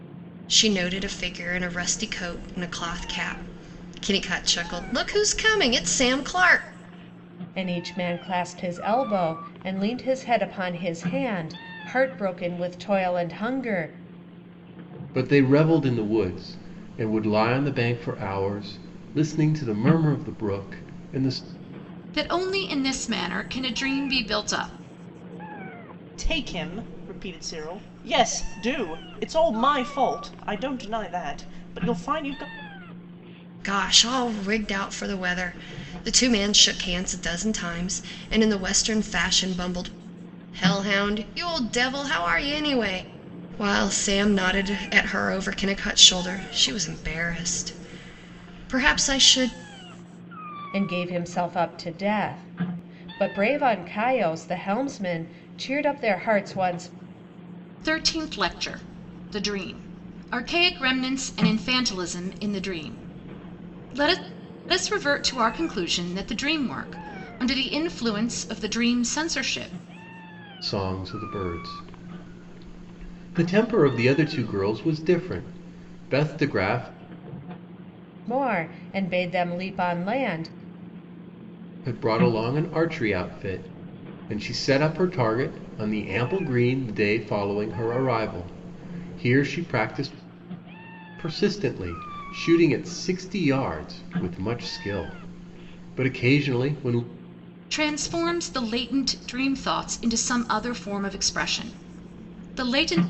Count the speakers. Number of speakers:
5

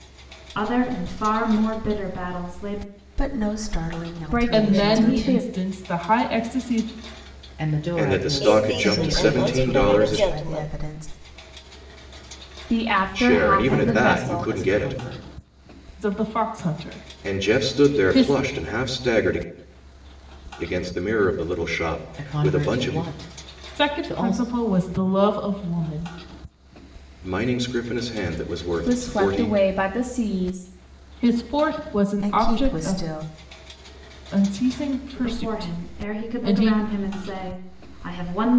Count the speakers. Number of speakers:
7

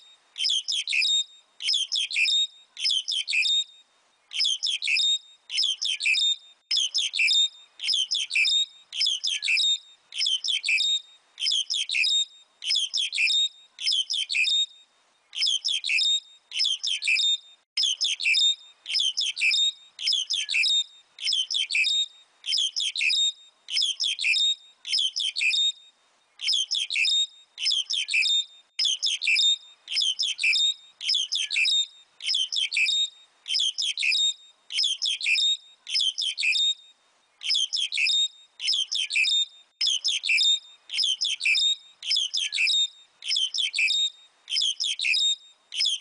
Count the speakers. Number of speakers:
0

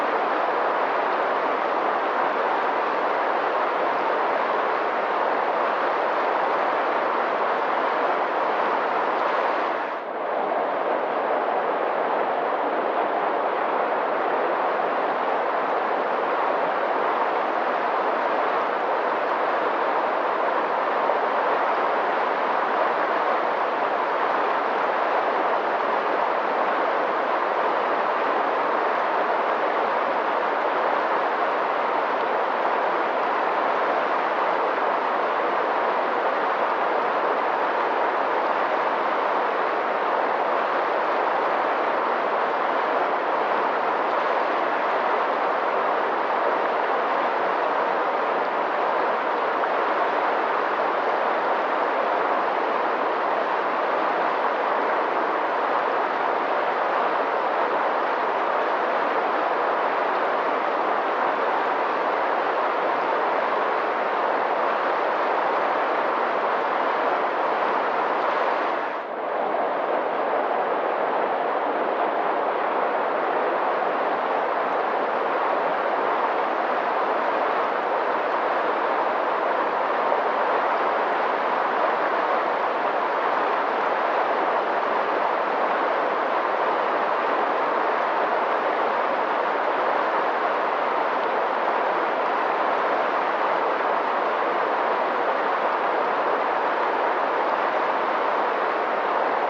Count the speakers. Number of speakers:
0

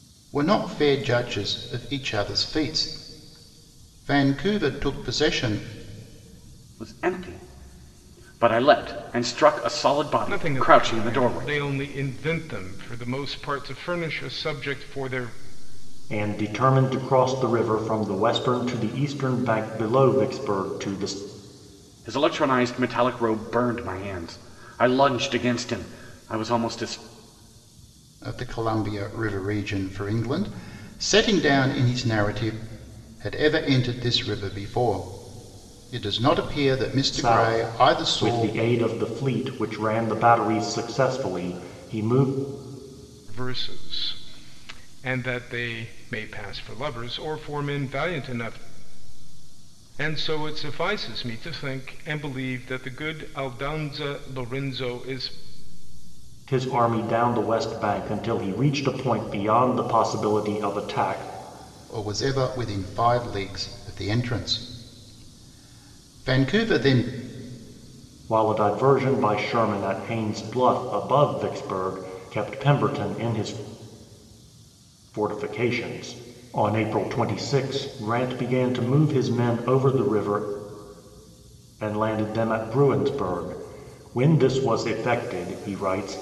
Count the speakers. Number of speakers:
4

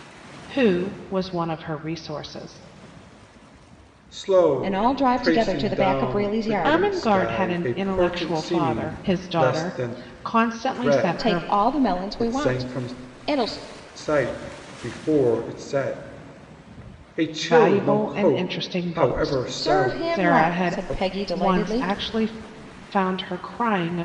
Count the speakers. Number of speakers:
3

